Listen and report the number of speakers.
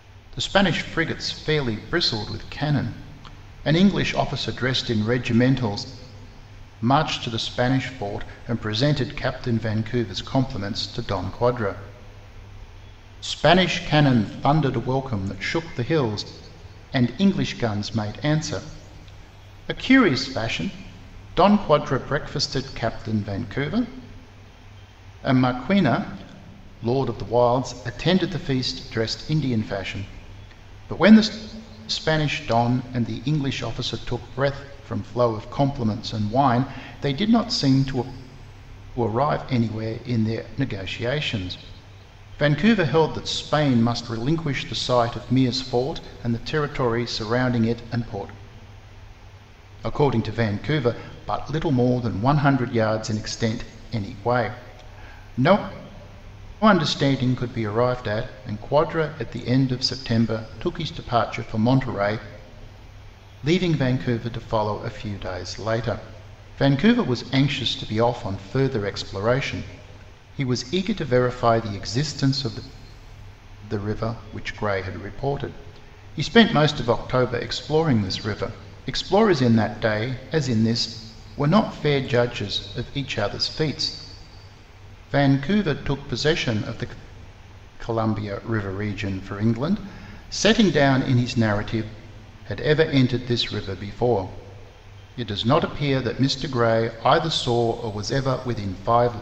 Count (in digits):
1